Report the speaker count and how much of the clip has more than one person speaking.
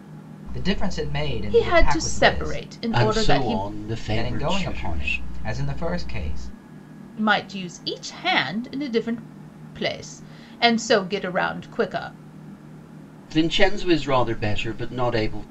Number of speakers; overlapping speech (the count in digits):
3, about 20%